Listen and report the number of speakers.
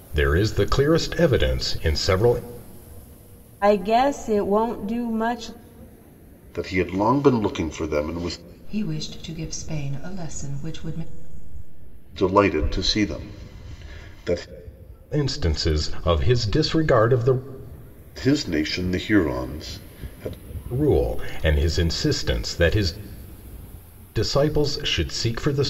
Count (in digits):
4